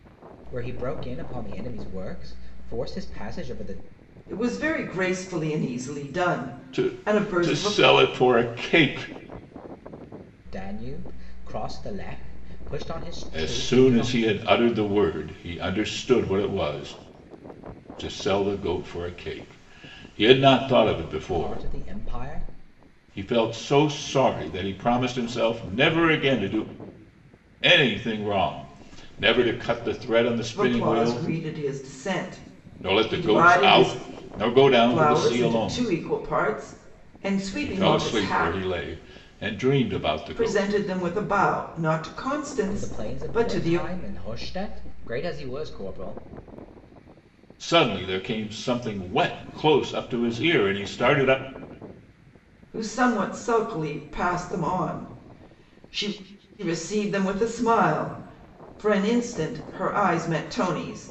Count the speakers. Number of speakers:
three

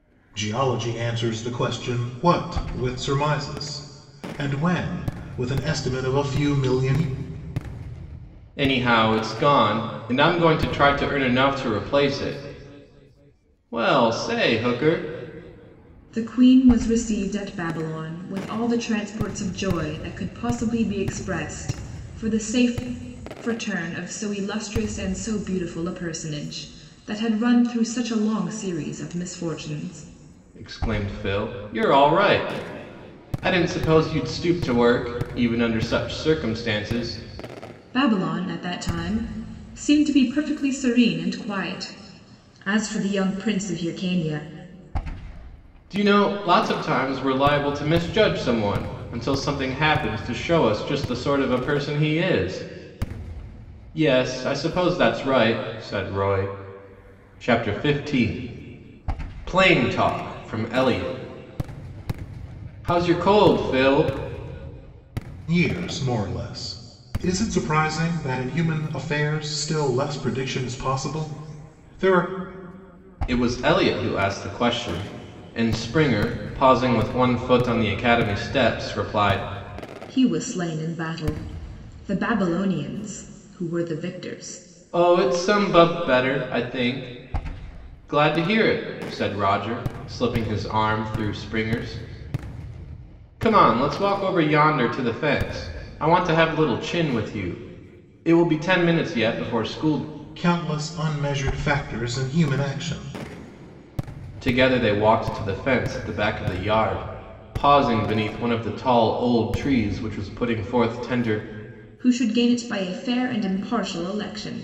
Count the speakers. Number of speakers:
three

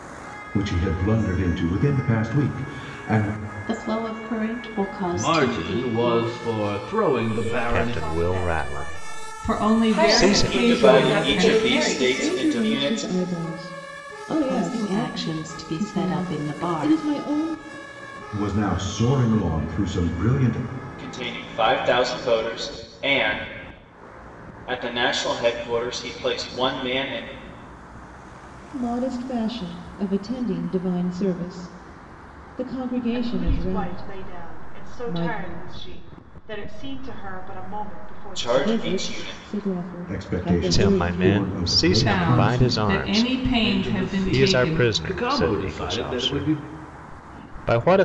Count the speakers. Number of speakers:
nine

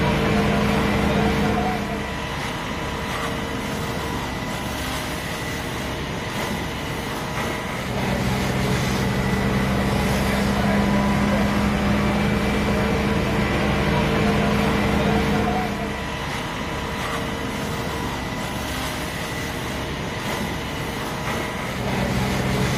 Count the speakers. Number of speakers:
zero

